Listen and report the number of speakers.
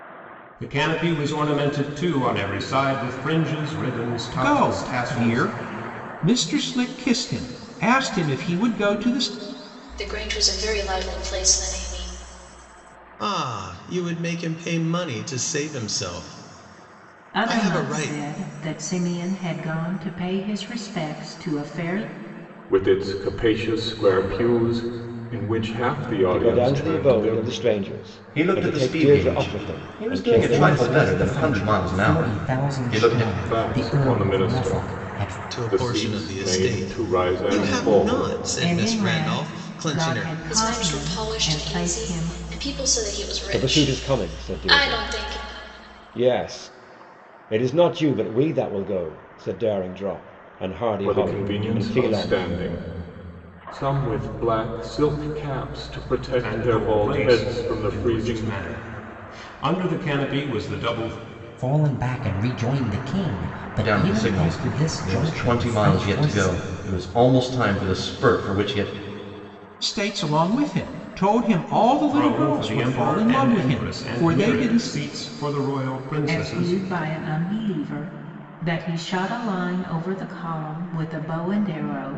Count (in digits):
9